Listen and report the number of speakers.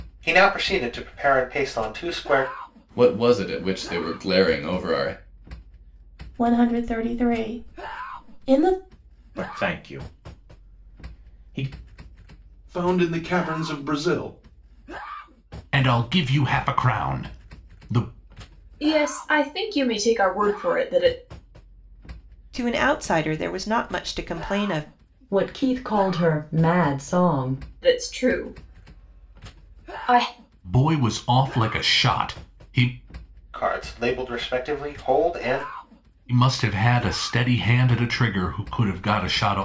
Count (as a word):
nine